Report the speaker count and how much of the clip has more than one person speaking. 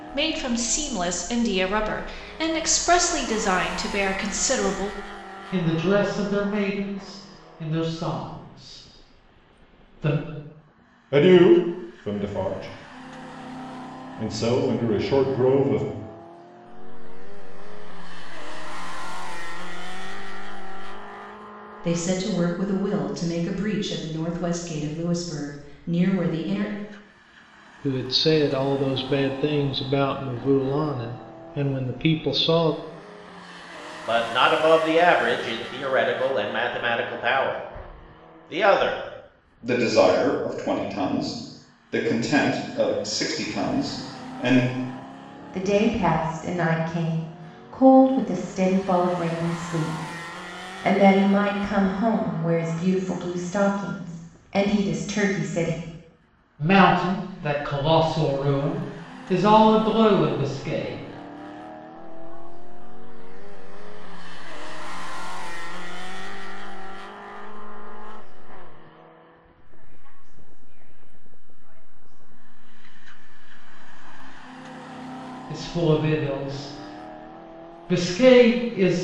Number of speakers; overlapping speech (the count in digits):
9, no overlap